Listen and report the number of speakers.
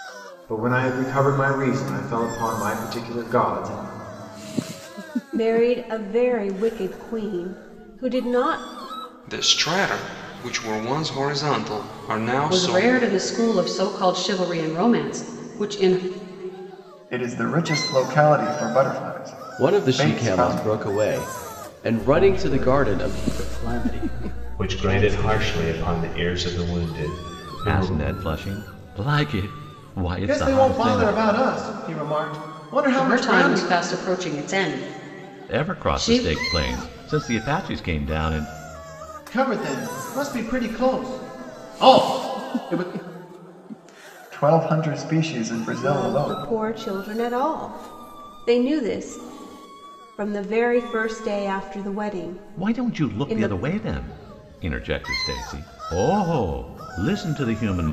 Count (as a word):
ten